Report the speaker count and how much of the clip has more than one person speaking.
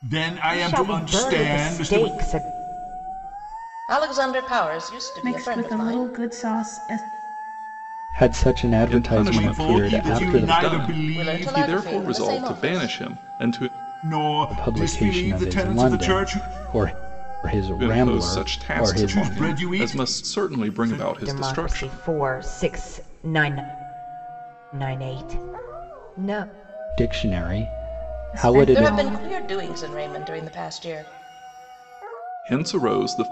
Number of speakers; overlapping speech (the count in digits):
6, about 41%